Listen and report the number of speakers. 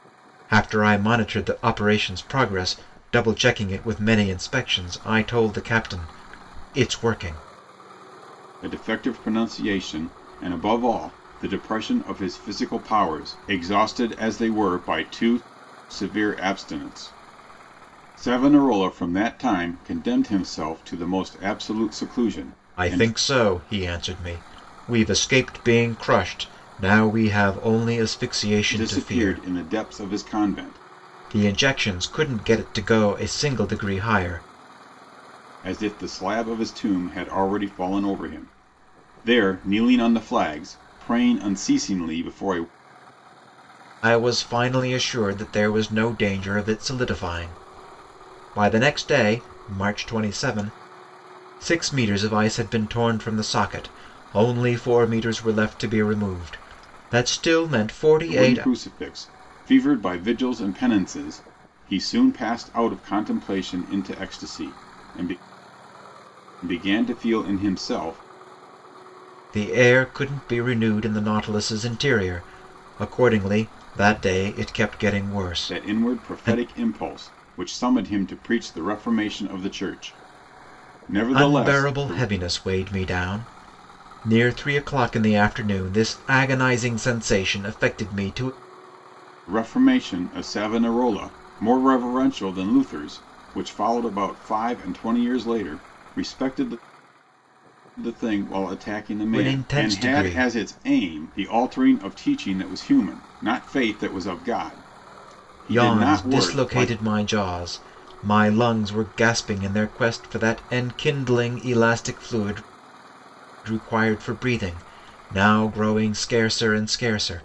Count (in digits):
2